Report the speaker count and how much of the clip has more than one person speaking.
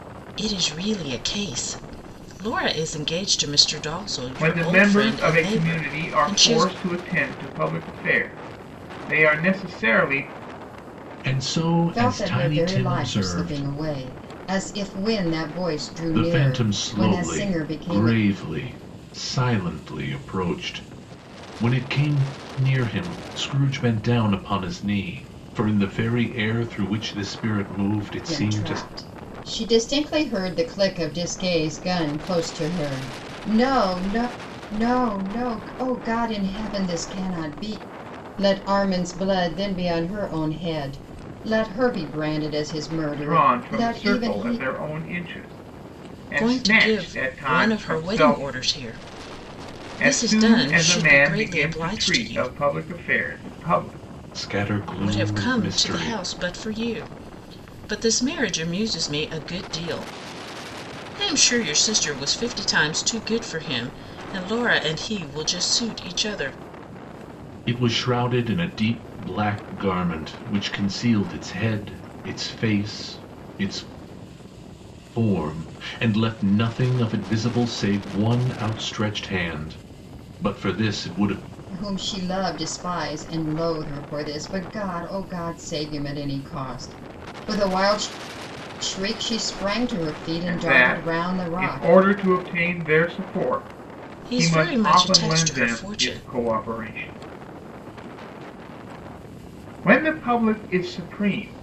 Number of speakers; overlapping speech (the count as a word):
four, about 18%